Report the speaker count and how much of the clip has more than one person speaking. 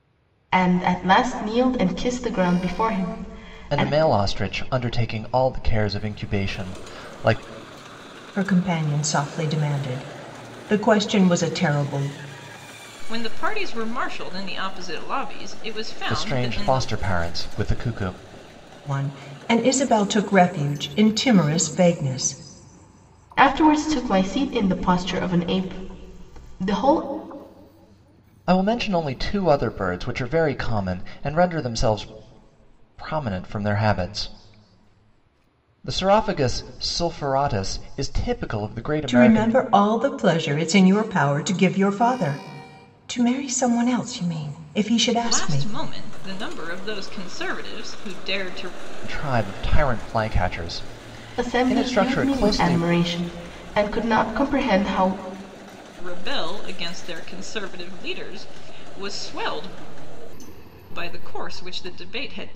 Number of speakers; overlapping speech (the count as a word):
four, about 6%